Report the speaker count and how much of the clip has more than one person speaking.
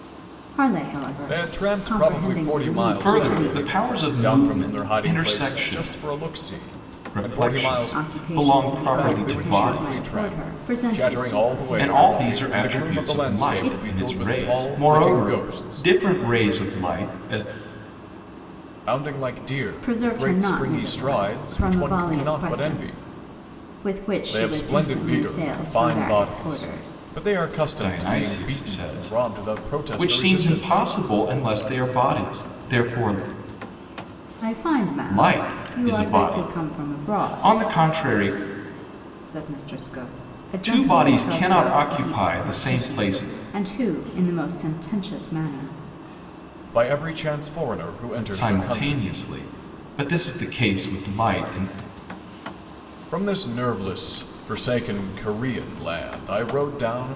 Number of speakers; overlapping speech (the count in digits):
3, about 50%